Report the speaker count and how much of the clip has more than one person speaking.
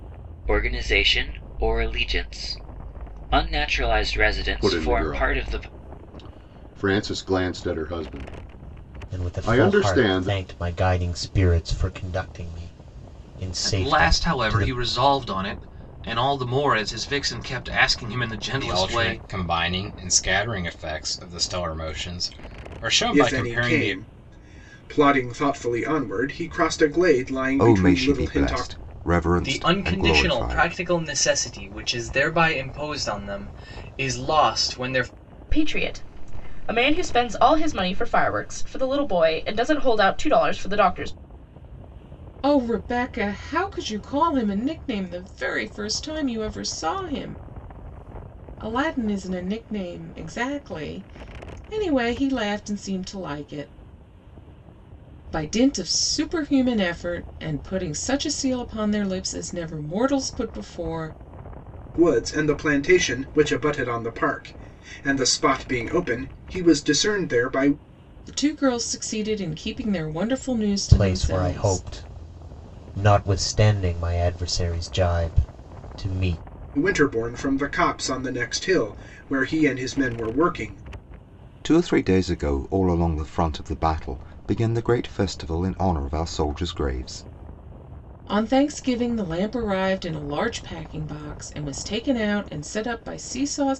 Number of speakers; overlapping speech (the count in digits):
10, about 9%